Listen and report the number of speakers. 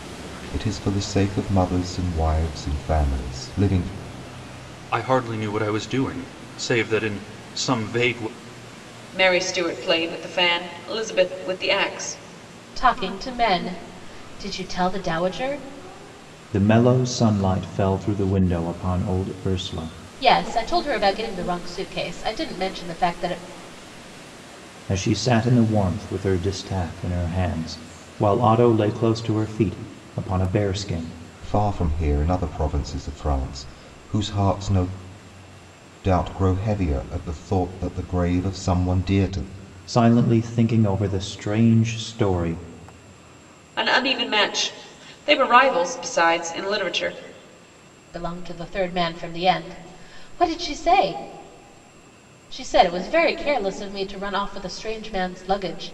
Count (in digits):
5